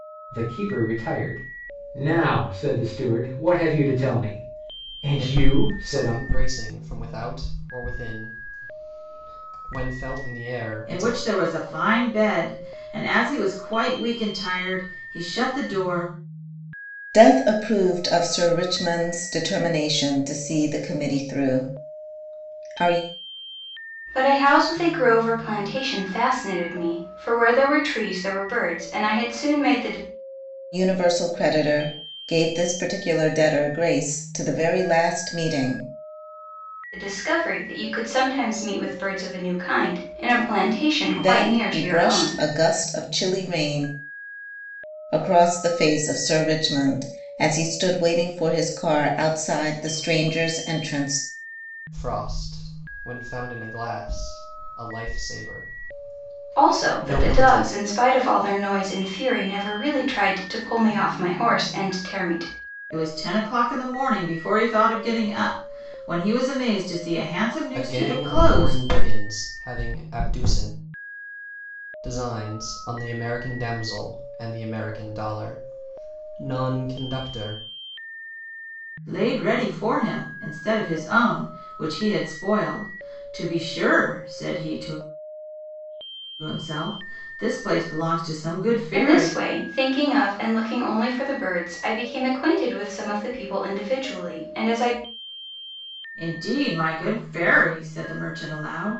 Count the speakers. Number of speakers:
5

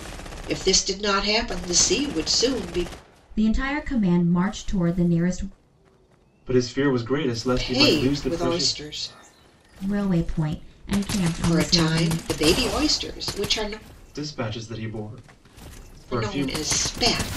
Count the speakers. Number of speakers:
3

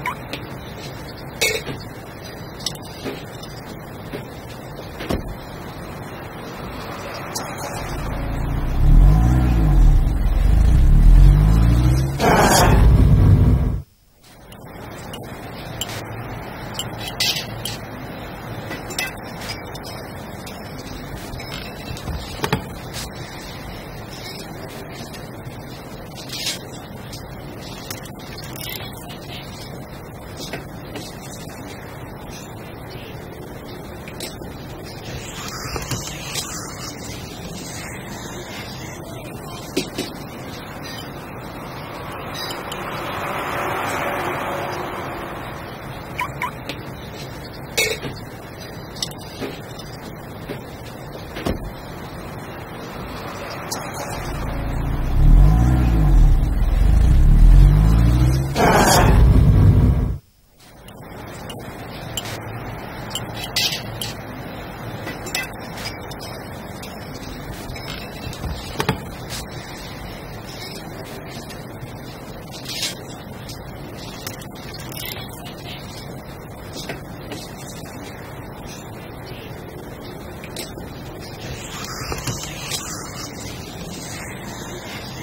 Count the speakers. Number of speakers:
0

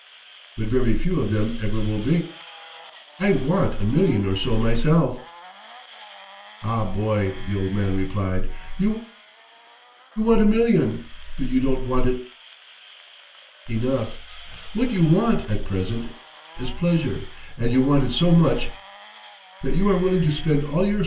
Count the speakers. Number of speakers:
1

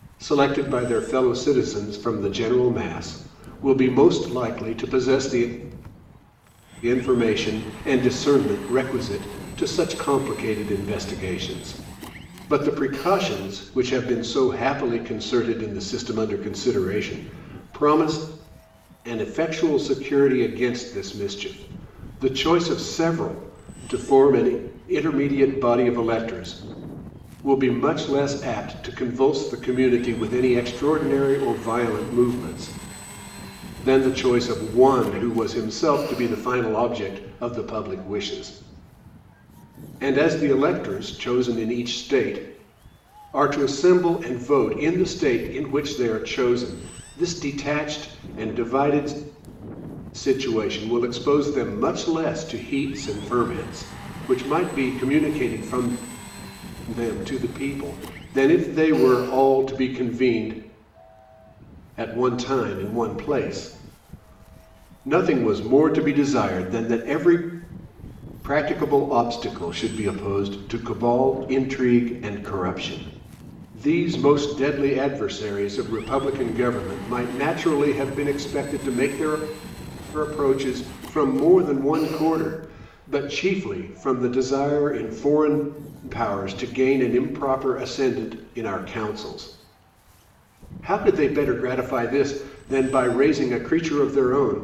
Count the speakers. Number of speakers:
1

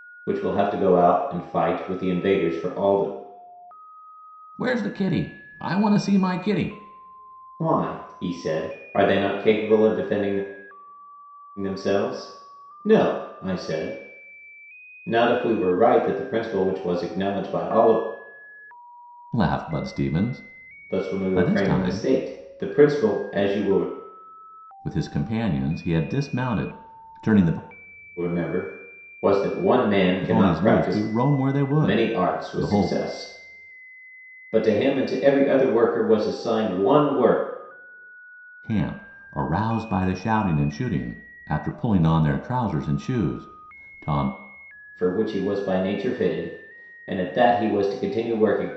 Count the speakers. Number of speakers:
2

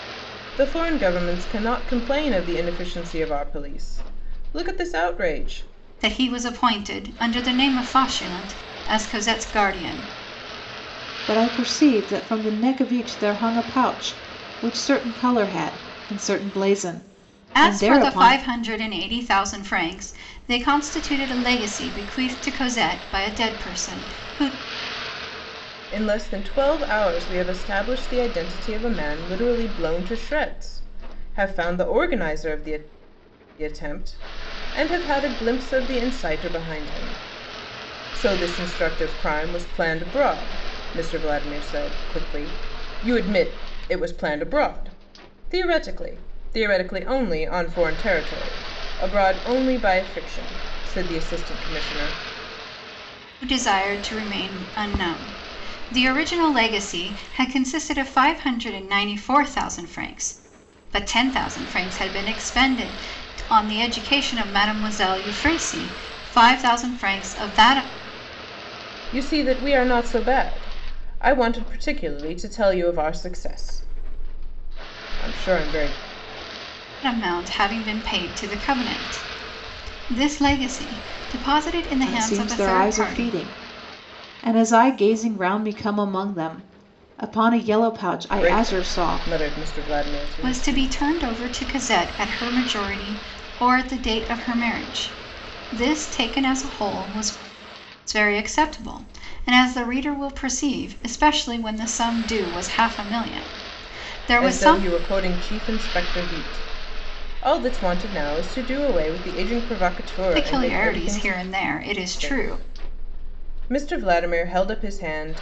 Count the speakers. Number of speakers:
3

